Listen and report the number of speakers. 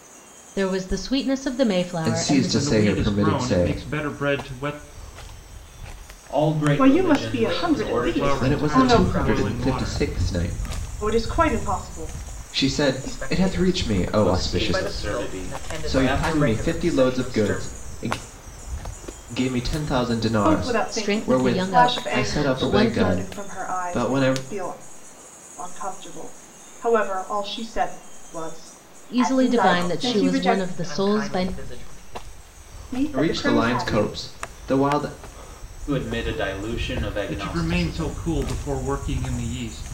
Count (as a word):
six